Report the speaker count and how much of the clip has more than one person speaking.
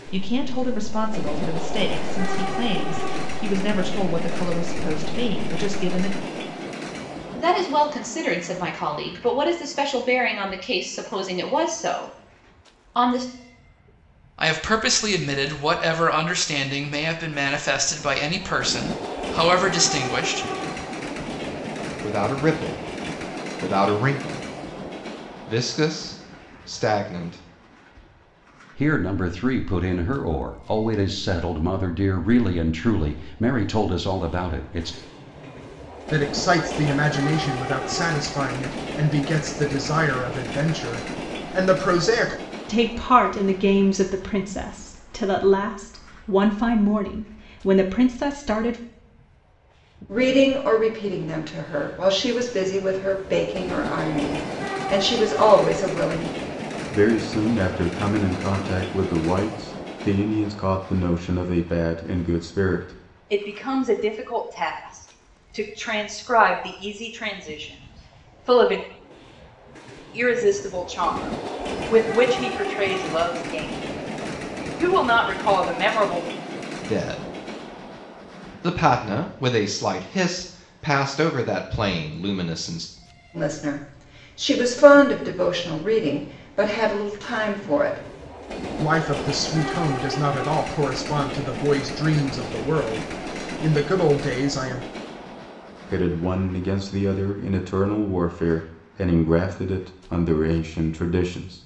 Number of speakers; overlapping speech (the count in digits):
10, no overlap